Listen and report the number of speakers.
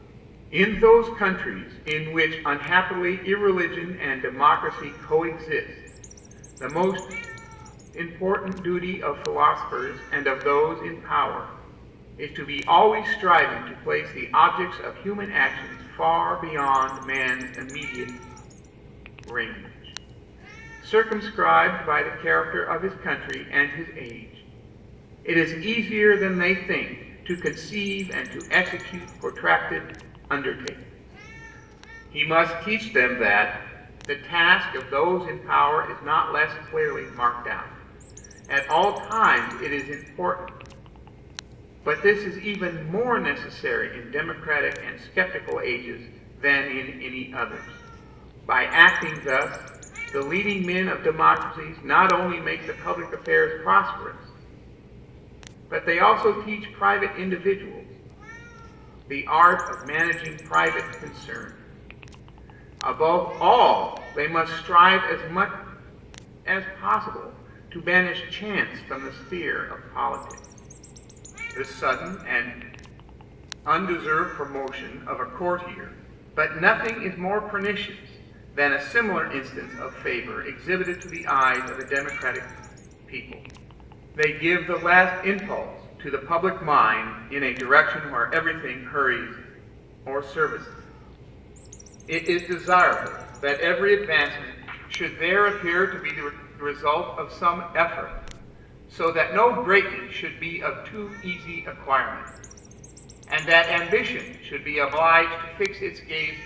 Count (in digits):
1